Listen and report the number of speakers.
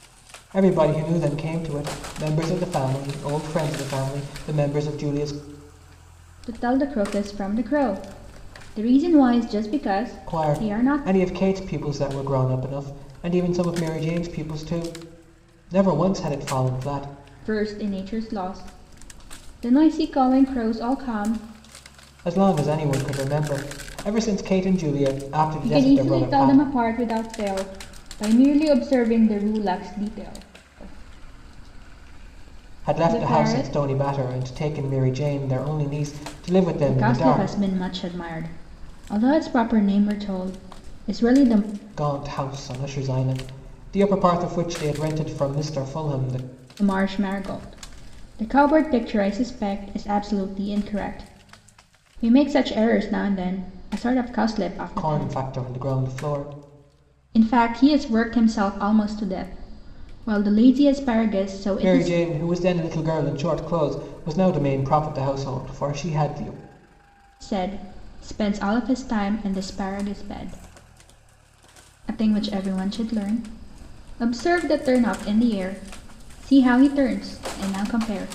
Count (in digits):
2